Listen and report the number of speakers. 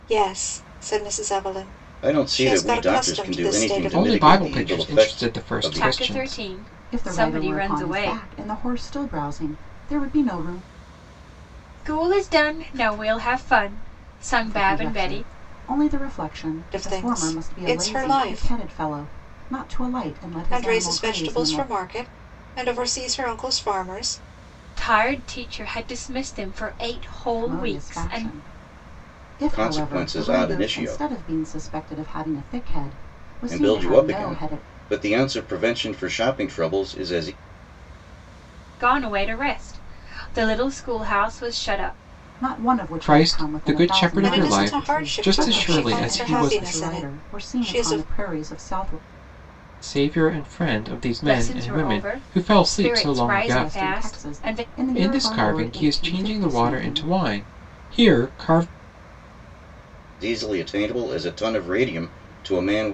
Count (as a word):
five